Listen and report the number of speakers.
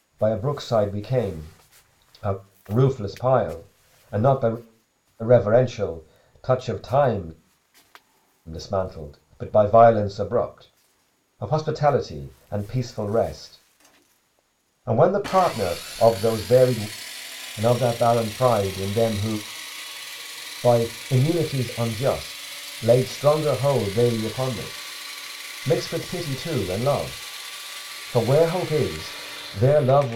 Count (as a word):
one